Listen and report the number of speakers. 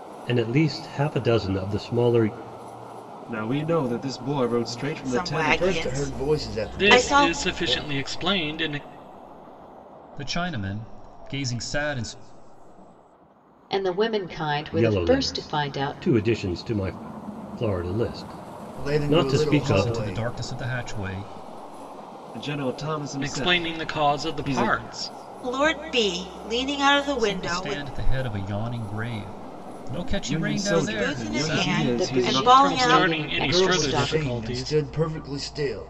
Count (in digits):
7